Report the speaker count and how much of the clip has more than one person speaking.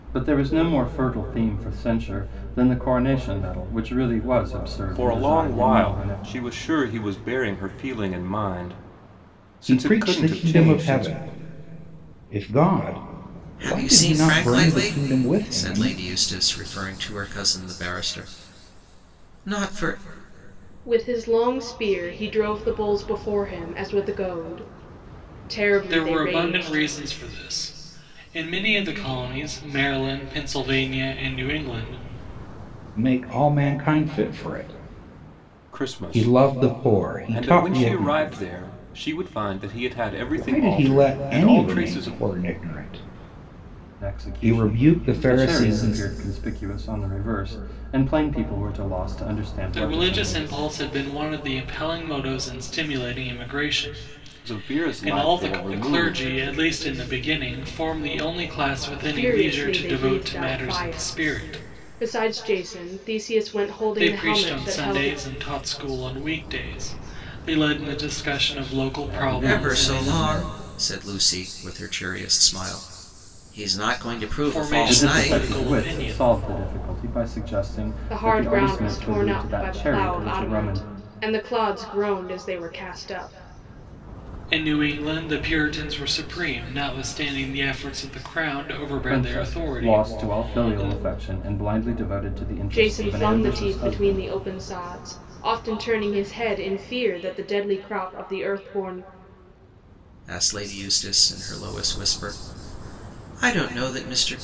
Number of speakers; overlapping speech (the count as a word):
six, about 28%